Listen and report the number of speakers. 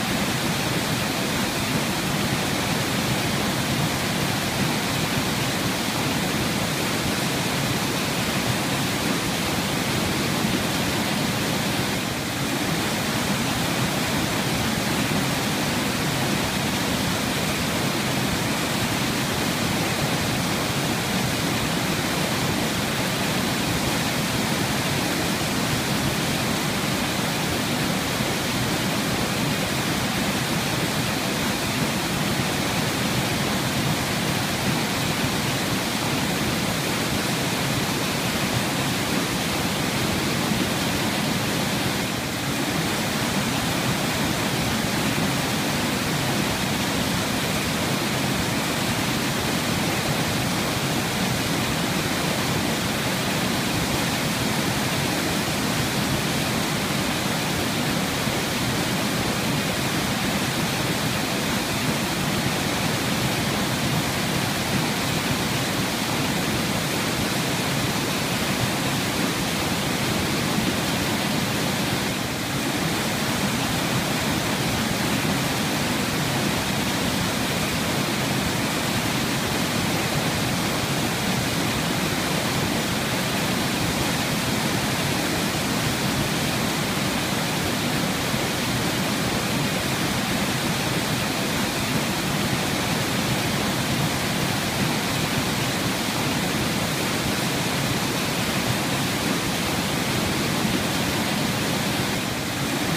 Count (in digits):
0